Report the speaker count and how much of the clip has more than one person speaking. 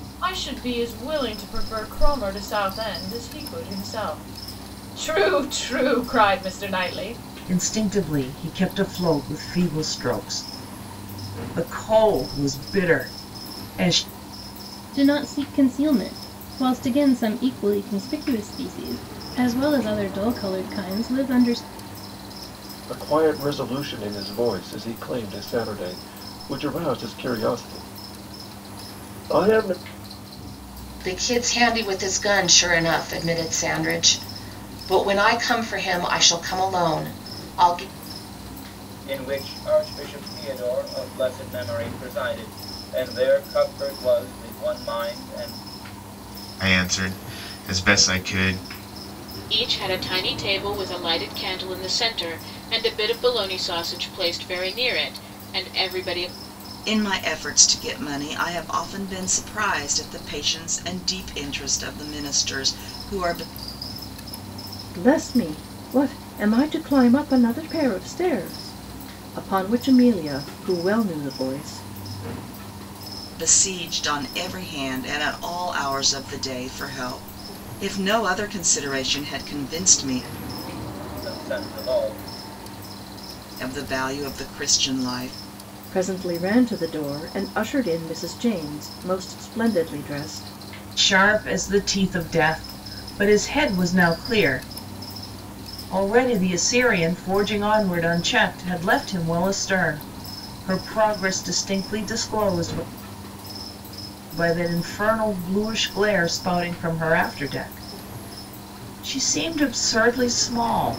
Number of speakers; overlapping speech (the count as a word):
ten, no overlap